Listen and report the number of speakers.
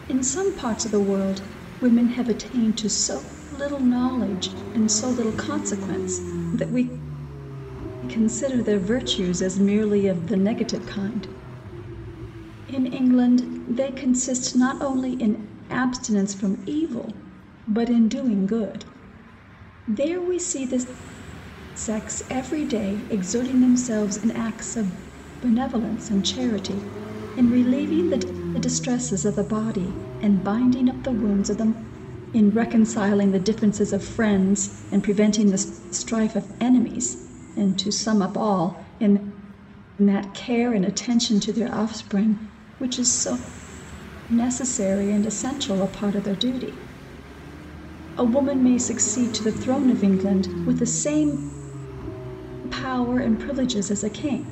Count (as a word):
one